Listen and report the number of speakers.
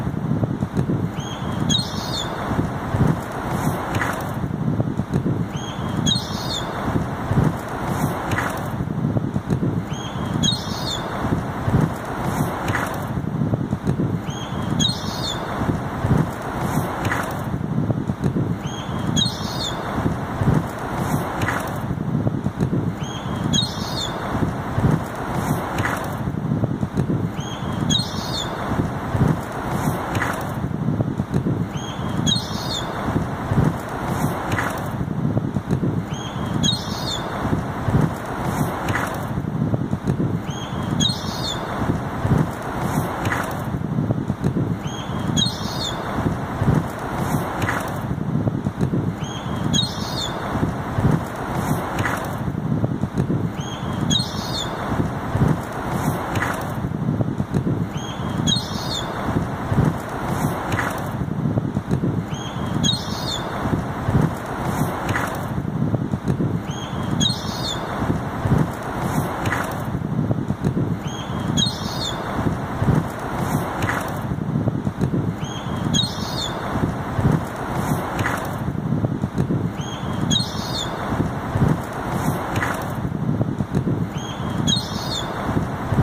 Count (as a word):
zero